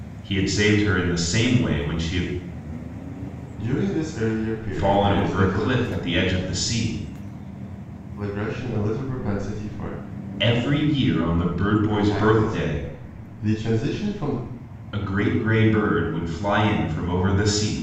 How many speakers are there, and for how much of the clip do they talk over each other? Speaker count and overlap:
two, about 11%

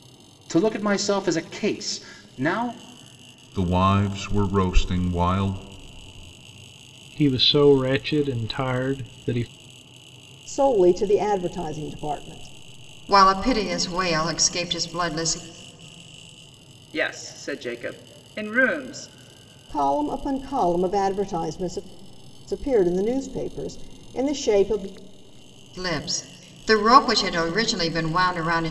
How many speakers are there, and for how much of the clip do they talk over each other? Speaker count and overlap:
six, no overlap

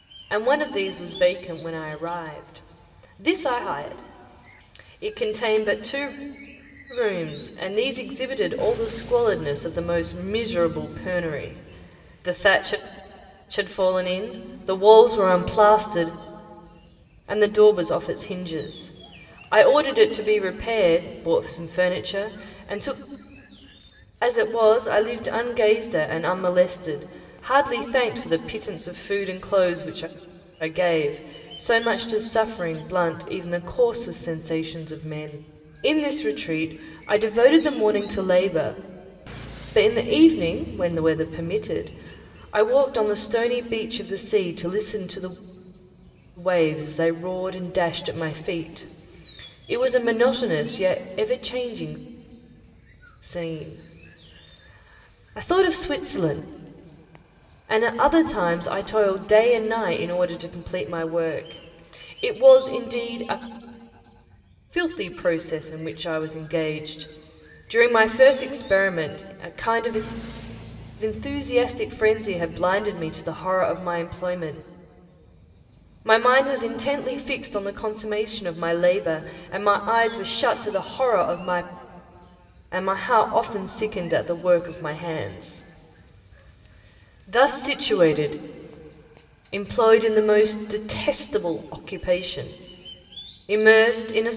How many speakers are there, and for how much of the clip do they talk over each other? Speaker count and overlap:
one, no overlap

